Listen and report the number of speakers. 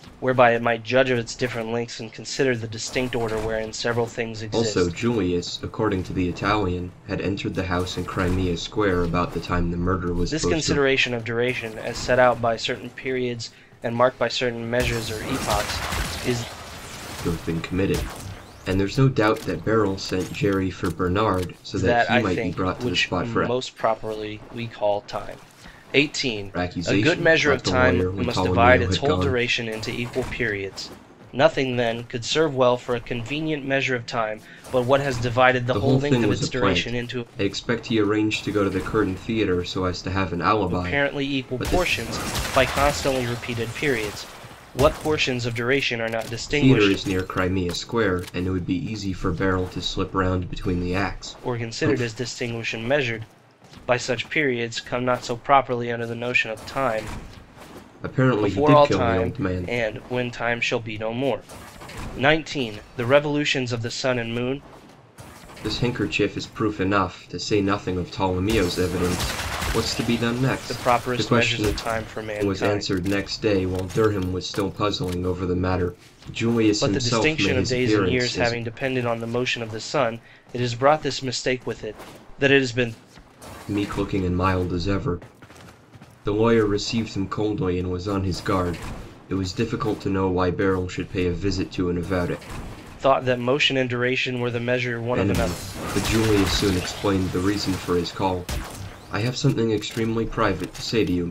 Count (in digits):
2